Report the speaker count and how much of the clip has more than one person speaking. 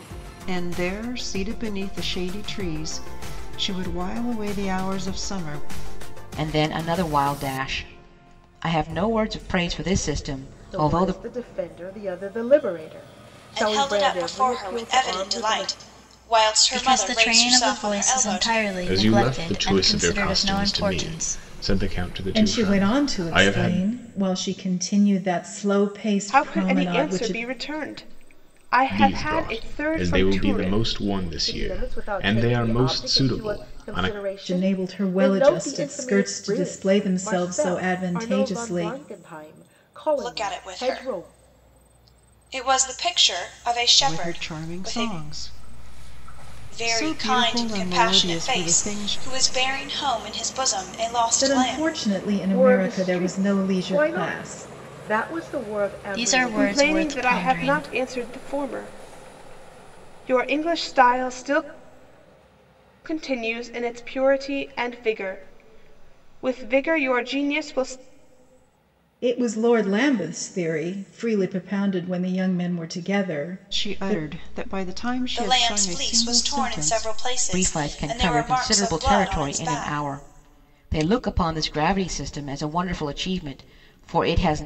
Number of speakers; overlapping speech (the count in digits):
8, about 40%